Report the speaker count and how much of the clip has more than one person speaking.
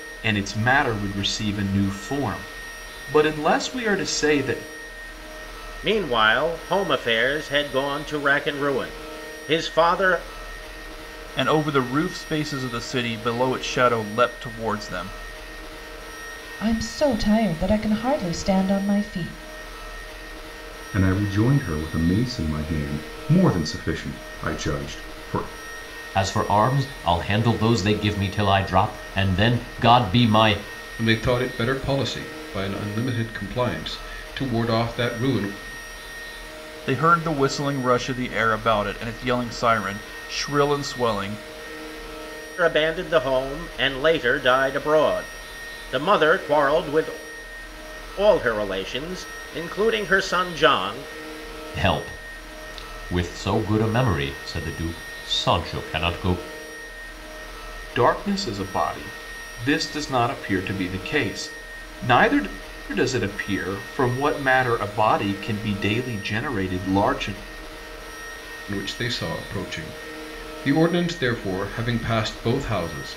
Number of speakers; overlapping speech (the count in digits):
7, no overlap